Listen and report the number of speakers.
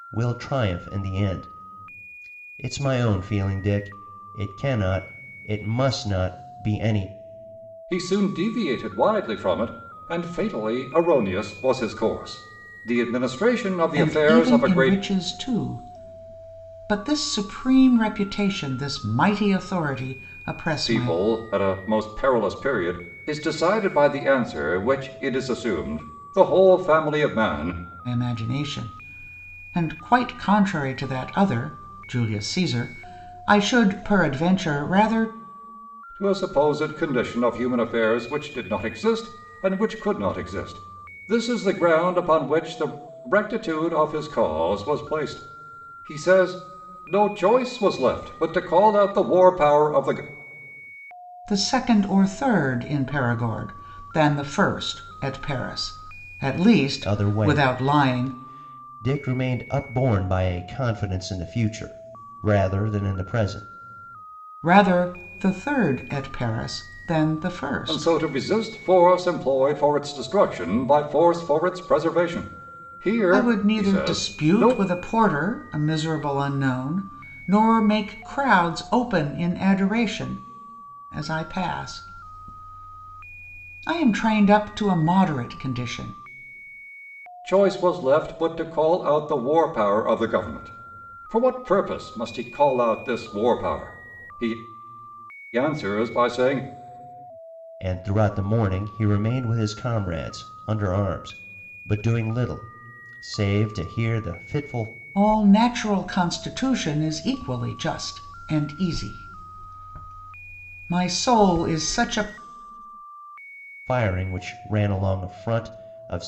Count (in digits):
3